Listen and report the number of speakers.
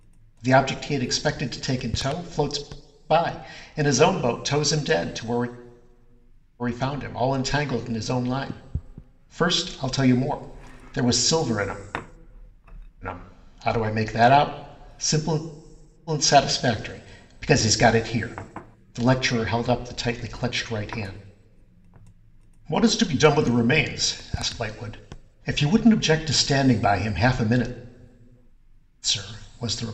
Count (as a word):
one